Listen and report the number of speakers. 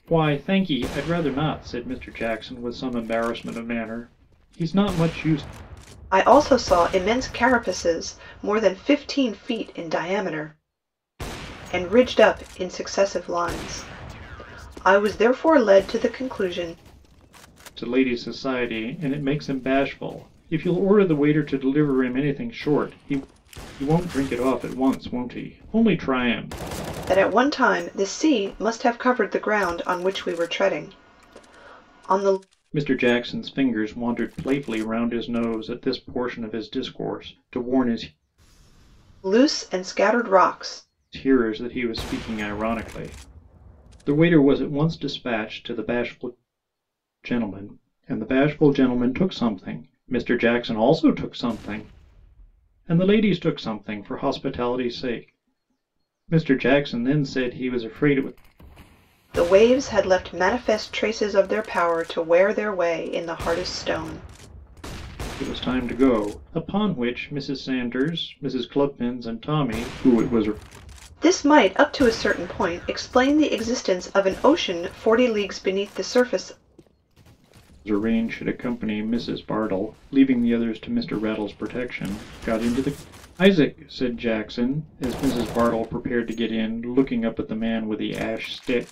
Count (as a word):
two